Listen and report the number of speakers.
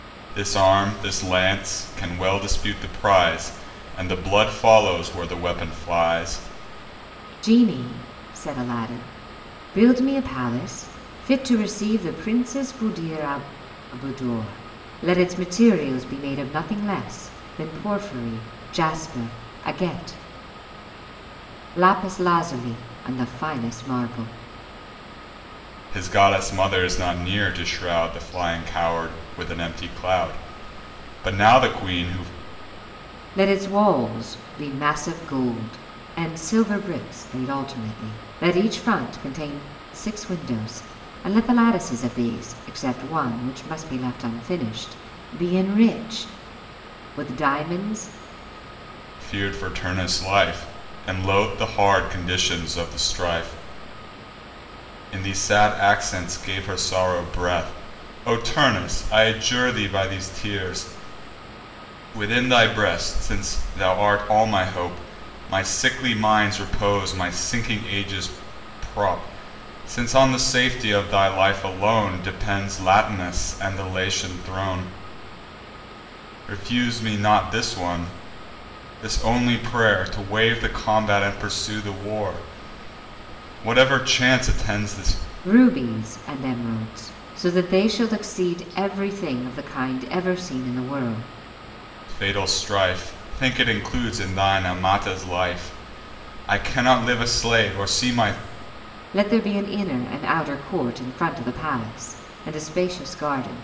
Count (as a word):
two